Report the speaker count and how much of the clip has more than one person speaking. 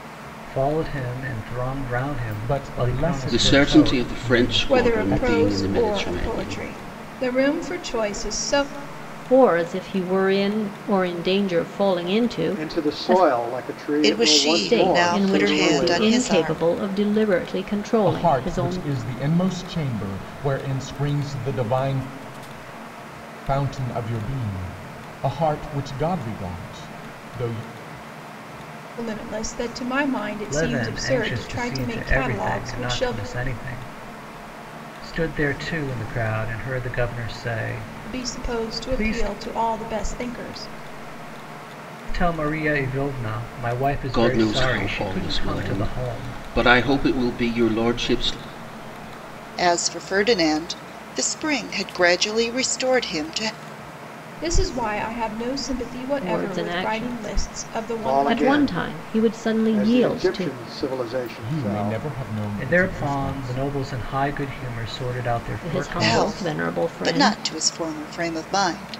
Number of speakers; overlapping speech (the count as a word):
seven, about 33%